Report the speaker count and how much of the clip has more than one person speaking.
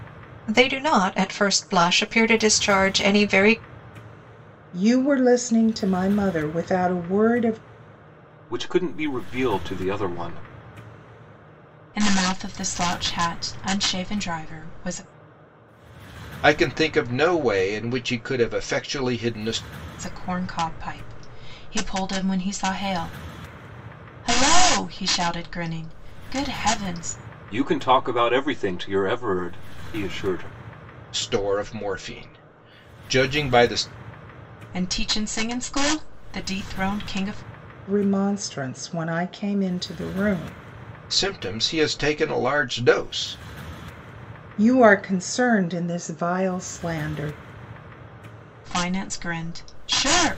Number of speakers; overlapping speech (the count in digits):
5, no overlap